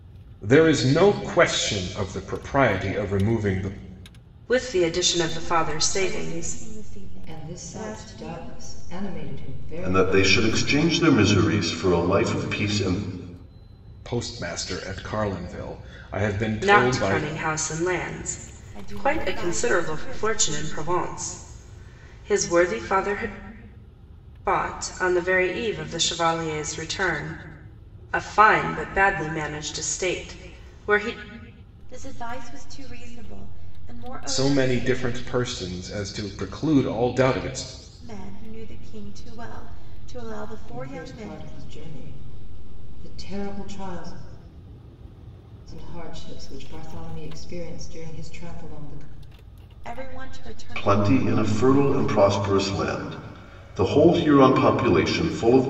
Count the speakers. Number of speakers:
5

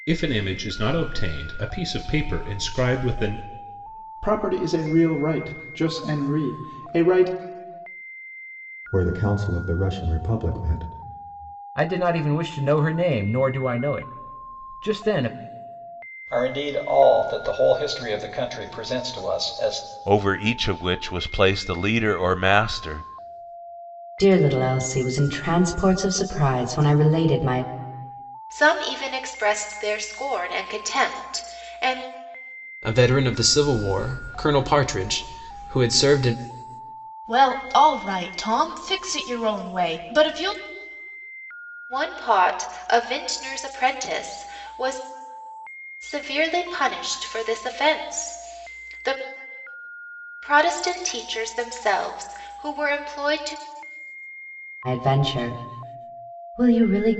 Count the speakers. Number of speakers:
10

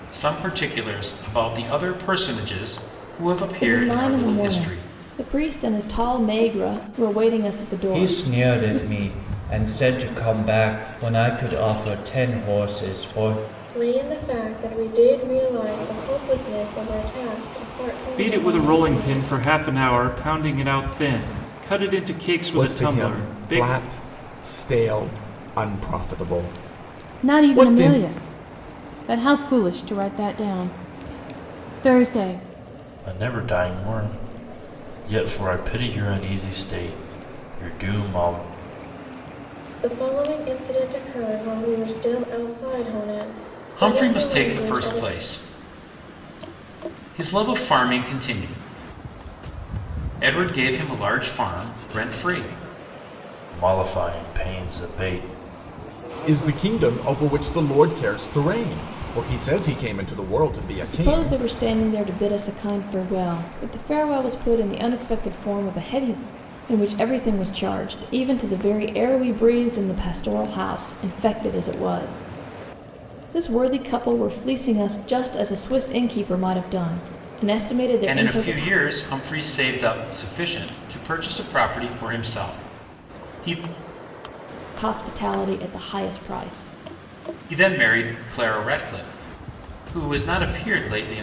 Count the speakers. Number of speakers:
8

